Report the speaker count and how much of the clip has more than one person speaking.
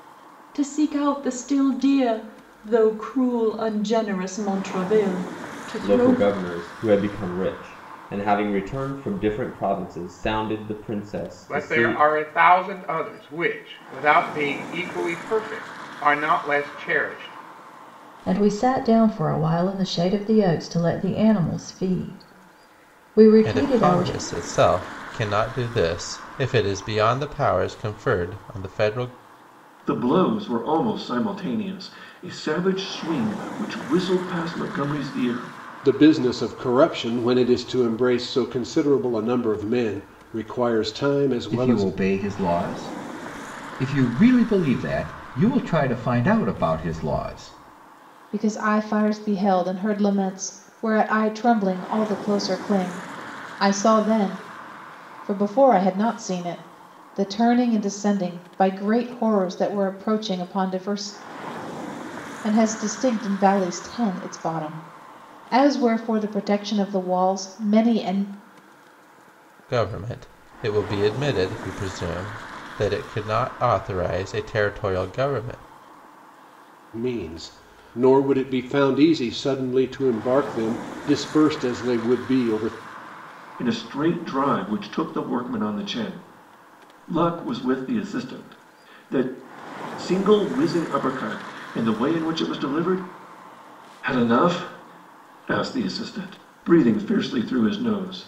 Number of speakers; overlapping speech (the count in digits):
9, about 2%